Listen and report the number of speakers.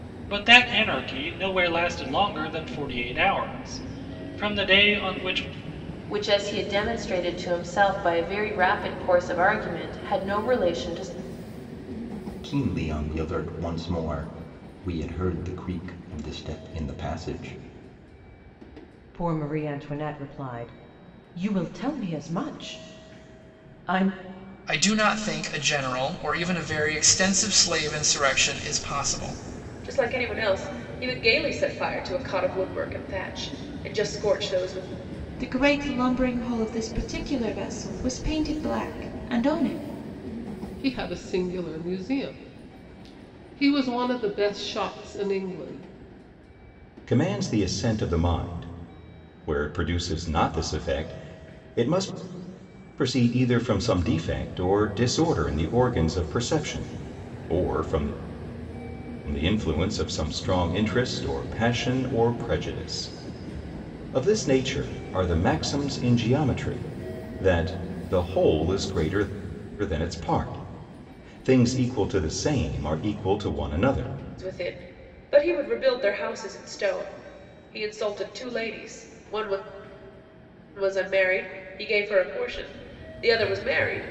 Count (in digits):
9